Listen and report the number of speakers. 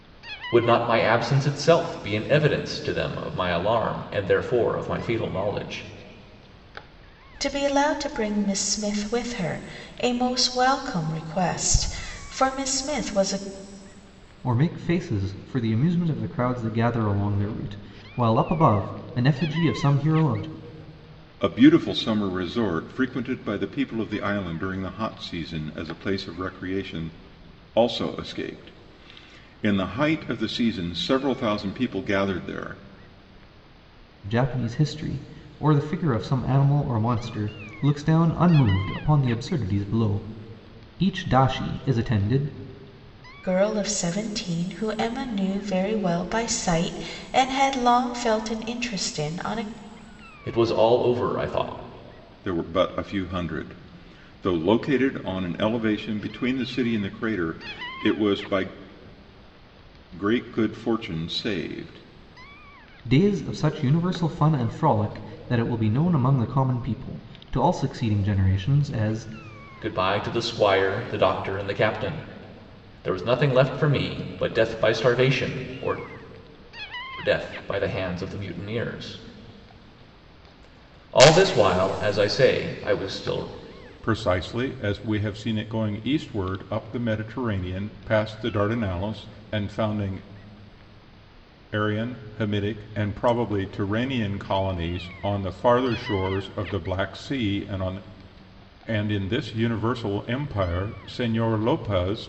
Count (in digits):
4